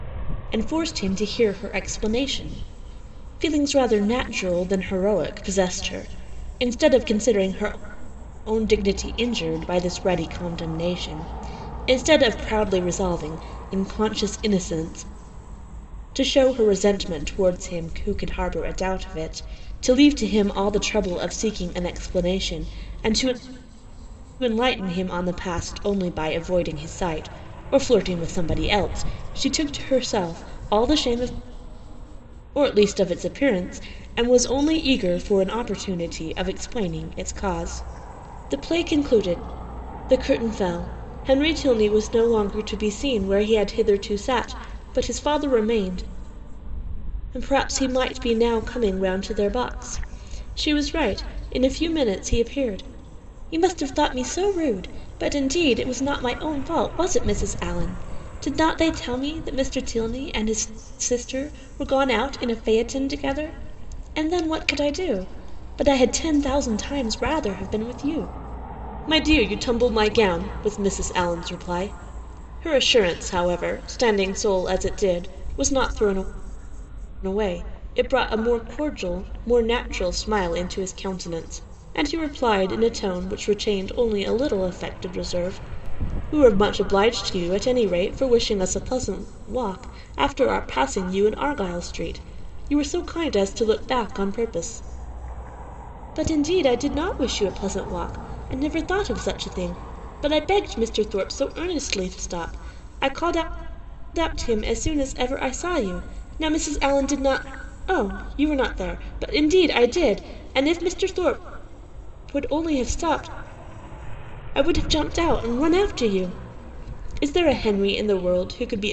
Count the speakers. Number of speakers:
1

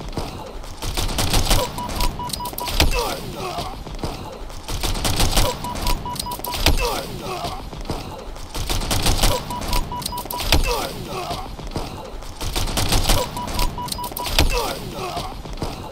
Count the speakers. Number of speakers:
0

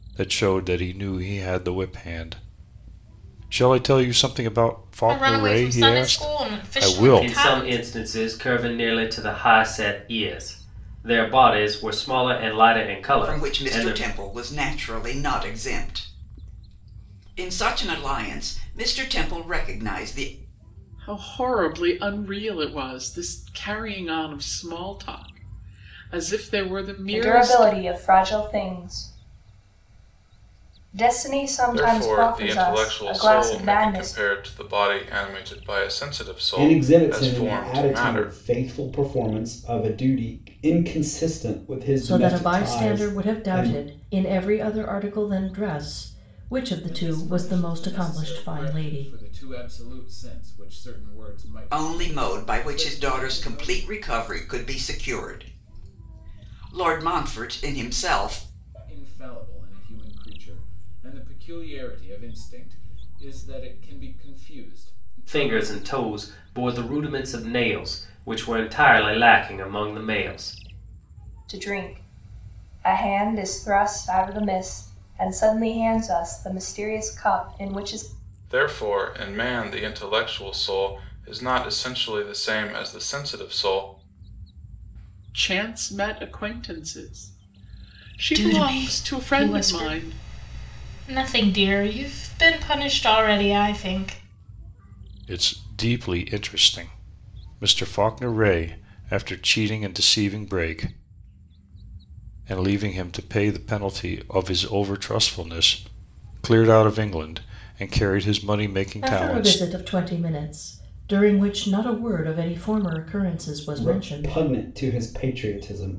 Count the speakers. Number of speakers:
10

